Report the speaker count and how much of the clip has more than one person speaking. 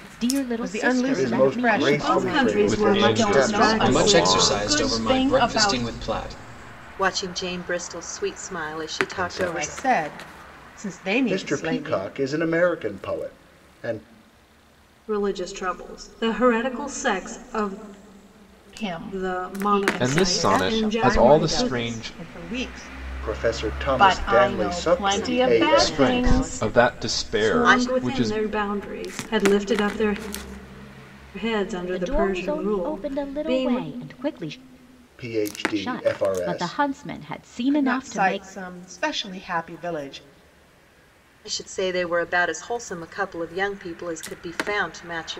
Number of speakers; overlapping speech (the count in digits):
8, about 41%